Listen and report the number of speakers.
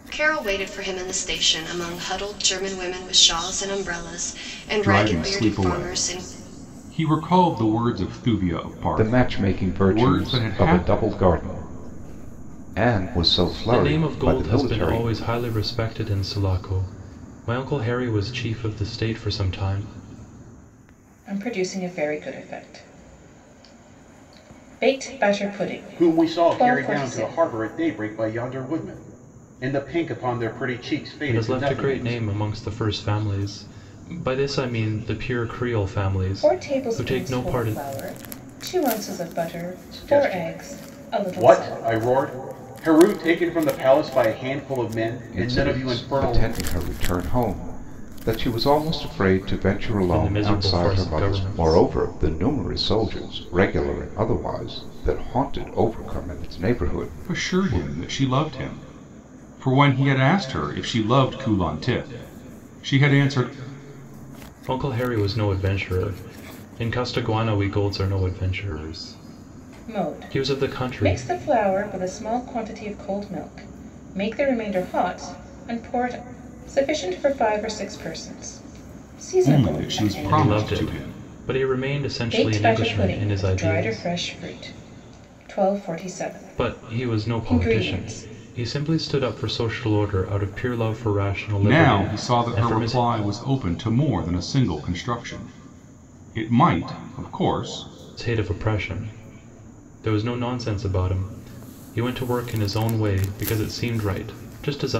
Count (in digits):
6